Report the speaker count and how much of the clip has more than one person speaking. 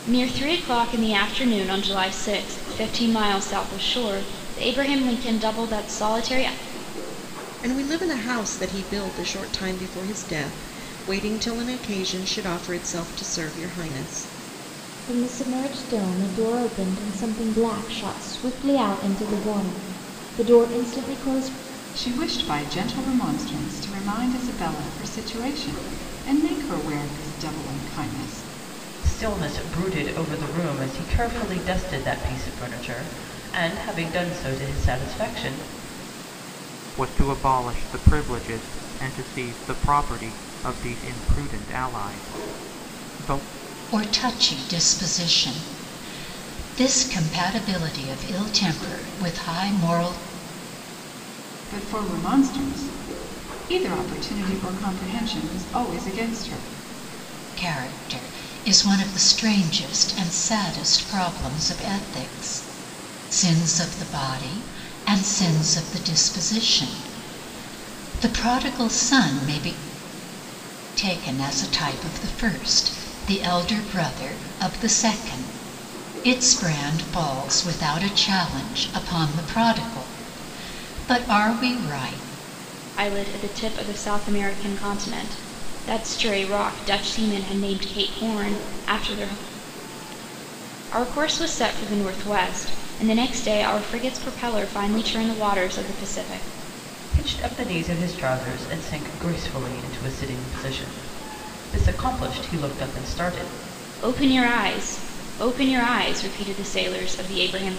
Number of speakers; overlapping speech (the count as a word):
seven, no overlap